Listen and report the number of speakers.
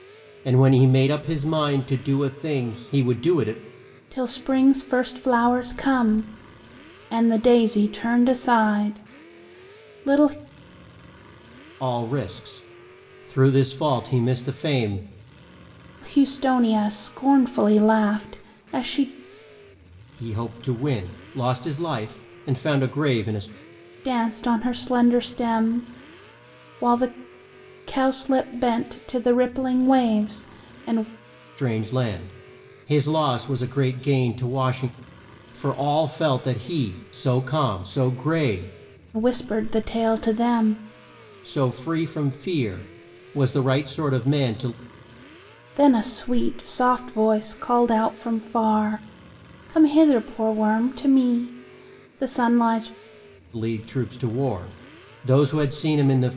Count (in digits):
2